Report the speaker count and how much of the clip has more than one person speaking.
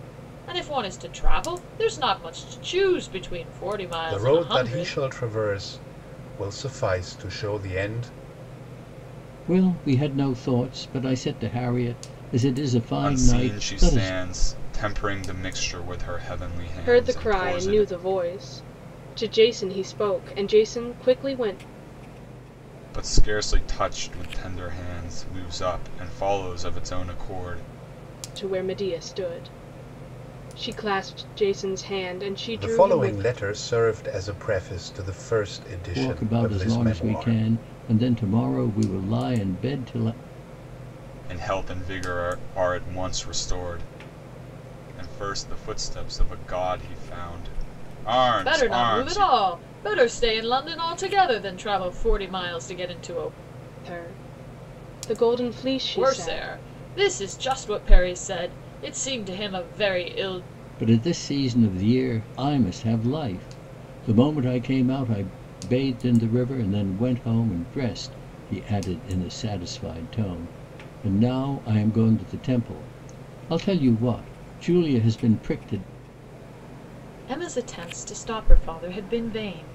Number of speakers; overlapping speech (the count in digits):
5, about 9%